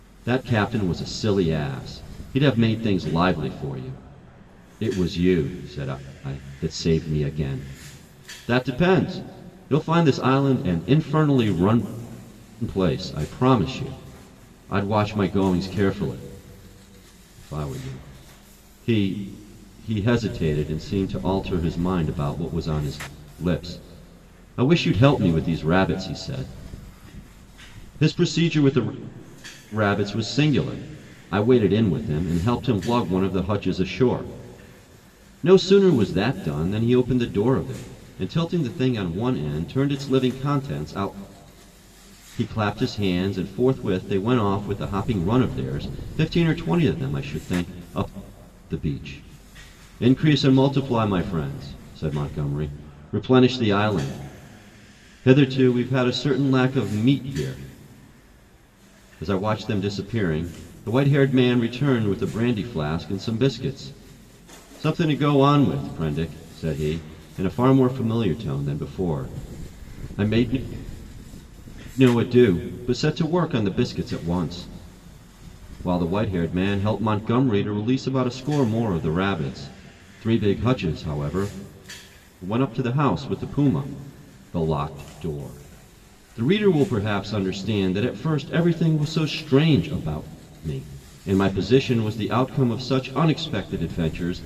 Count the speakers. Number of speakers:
one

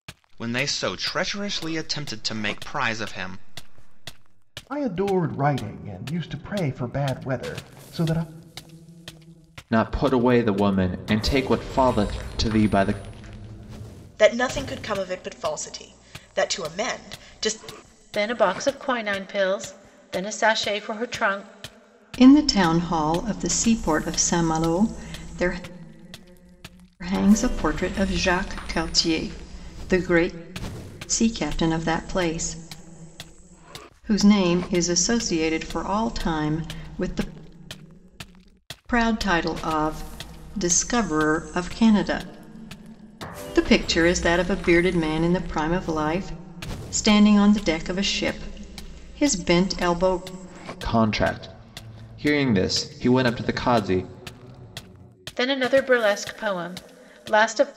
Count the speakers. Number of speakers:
six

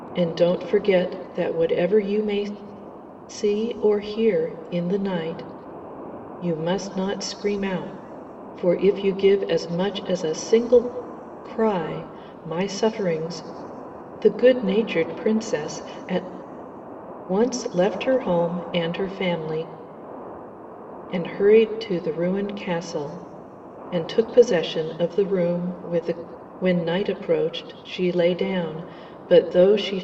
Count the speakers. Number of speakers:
one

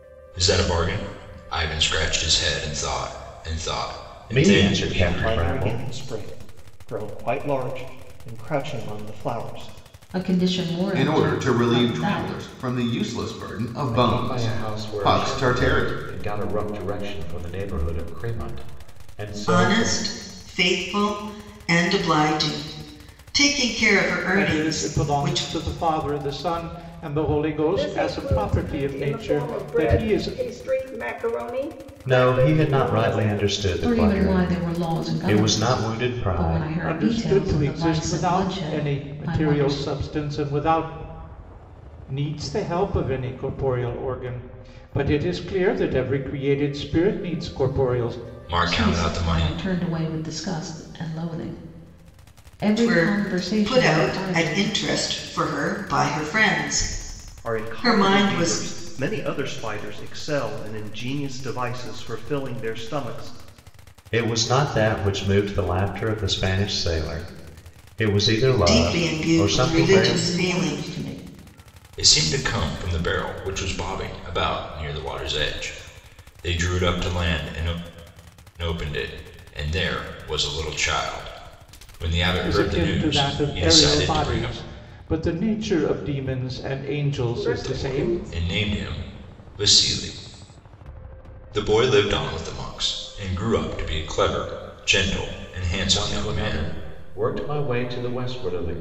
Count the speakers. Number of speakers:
nine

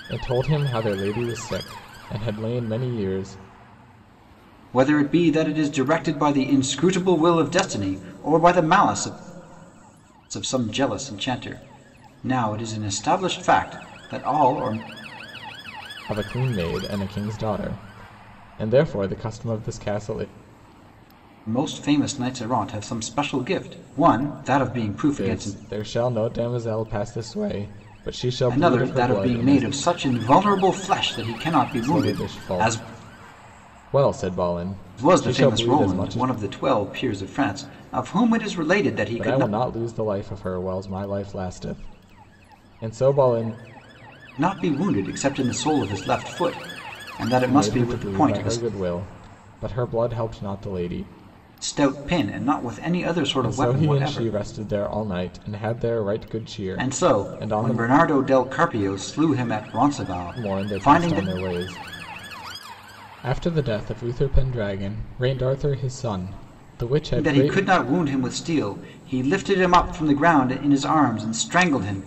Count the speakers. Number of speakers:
two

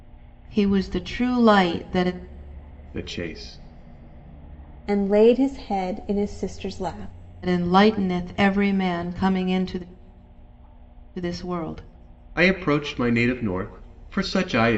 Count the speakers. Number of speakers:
three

